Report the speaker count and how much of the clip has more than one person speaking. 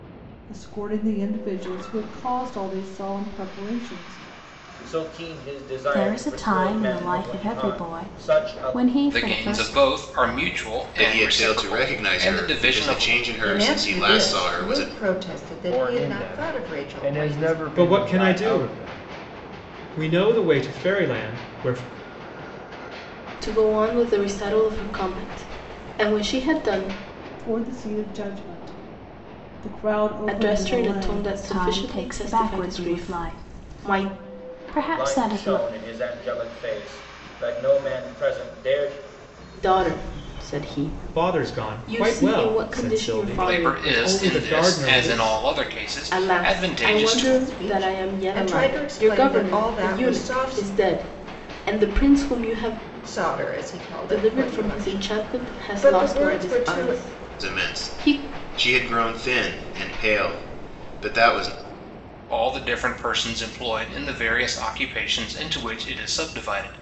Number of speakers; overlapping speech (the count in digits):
9, about 43%